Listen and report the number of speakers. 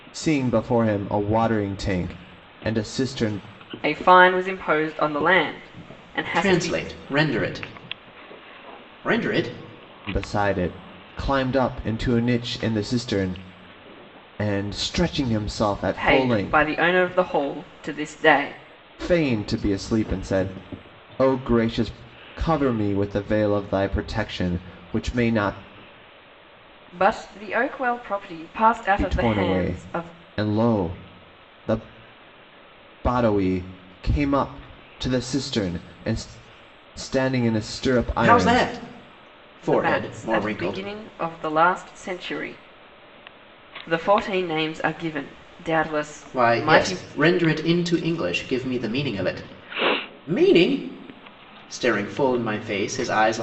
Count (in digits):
3